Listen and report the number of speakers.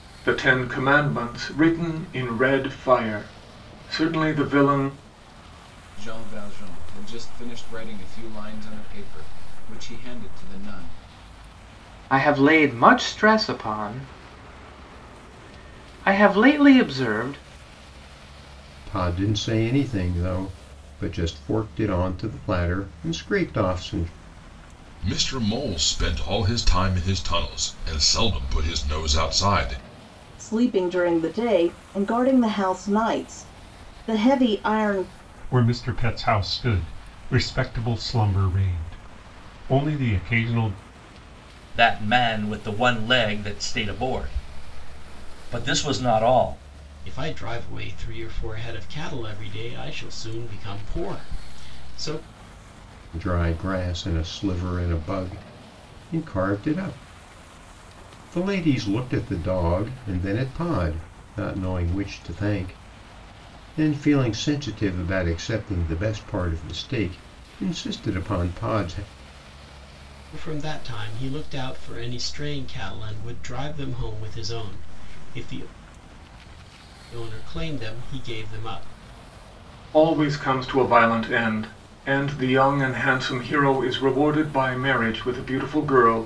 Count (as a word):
nine